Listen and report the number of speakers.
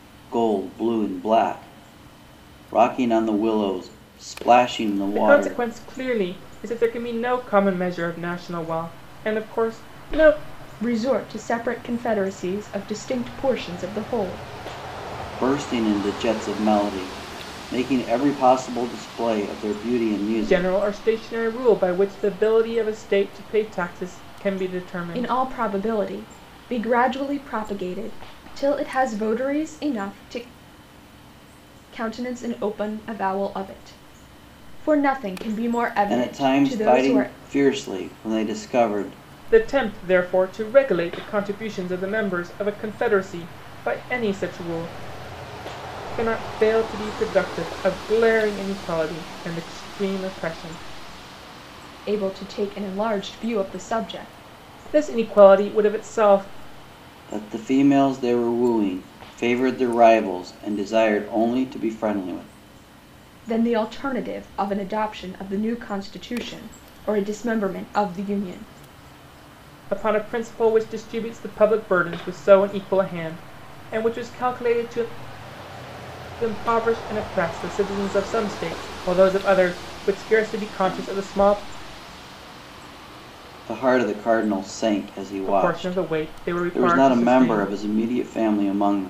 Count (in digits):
3